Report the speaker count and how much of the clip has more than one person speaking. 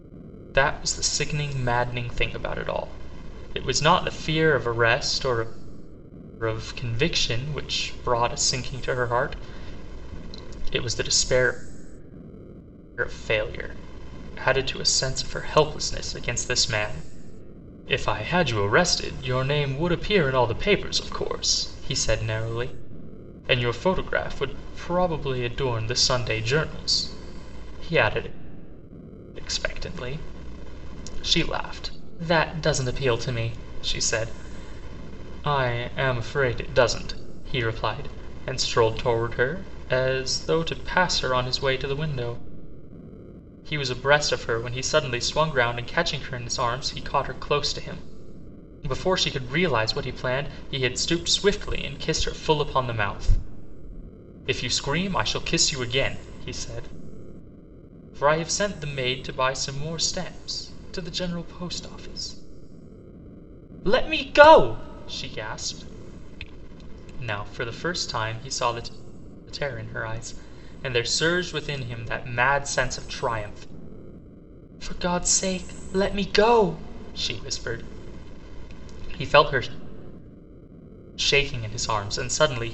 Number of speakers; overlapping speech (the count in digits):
1, no overlap